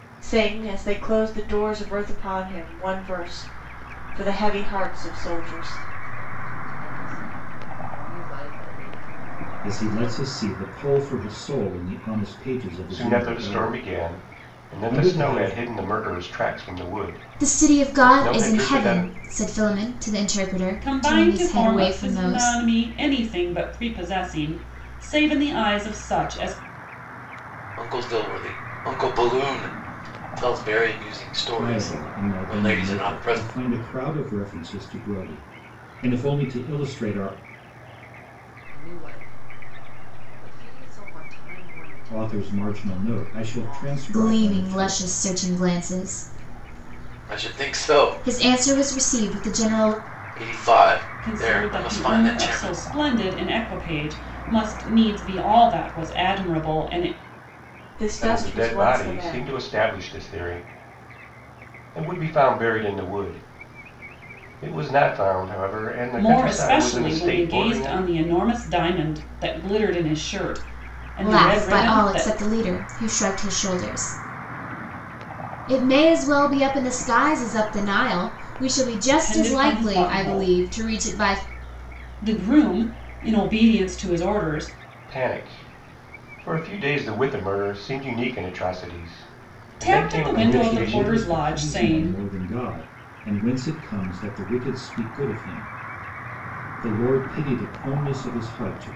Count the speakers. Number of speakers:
seven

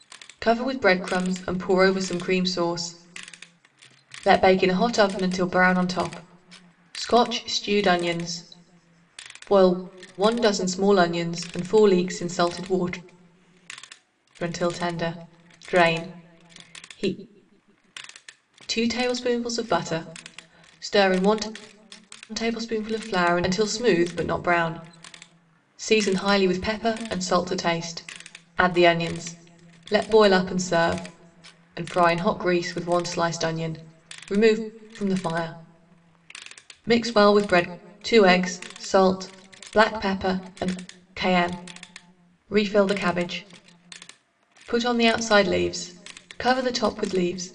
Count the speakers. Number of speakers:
one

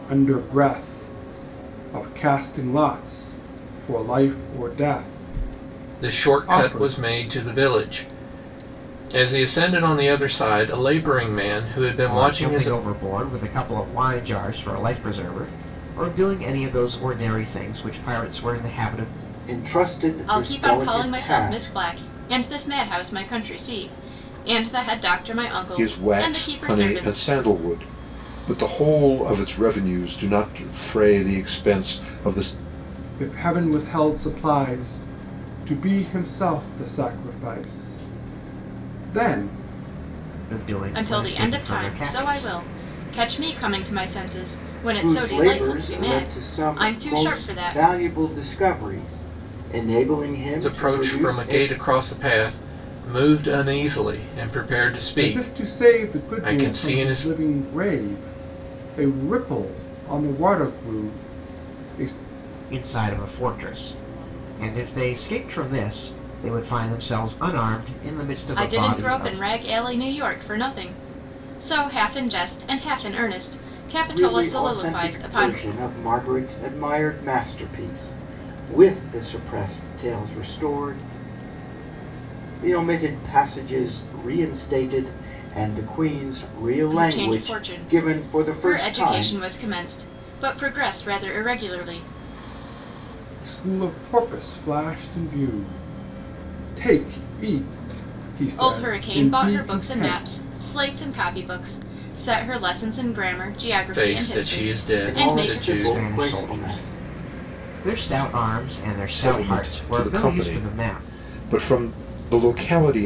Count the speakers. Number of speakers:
six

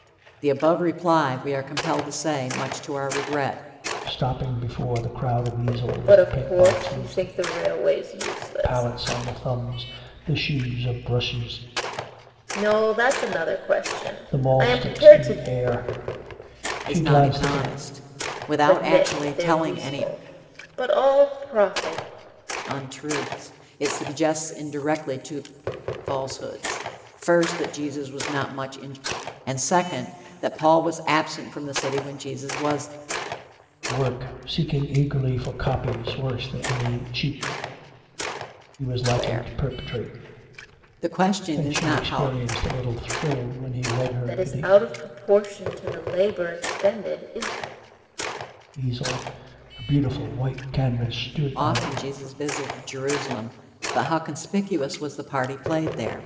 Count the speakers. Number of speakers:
three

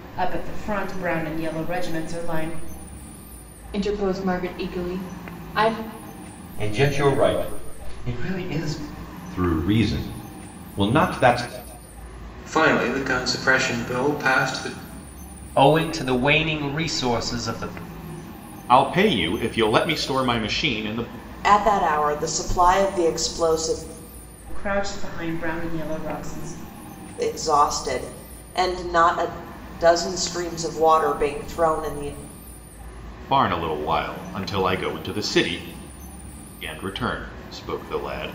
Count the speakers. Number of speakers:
eight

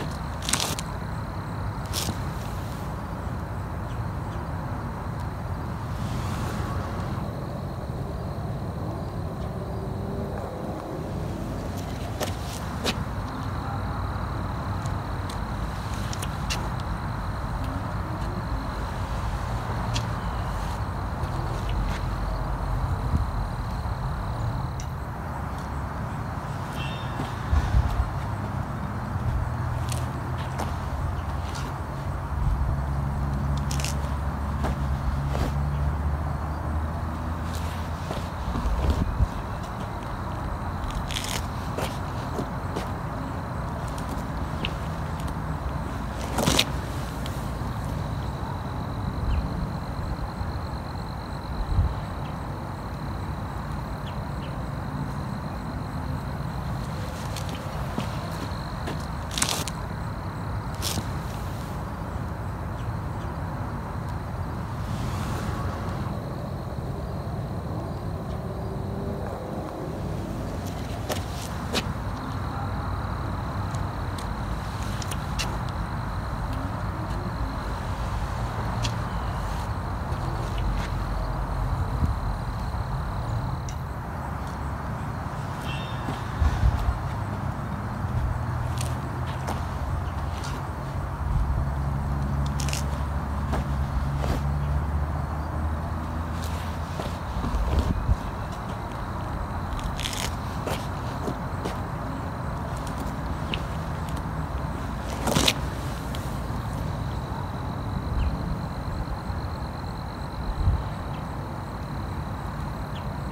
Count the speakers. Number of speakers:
zero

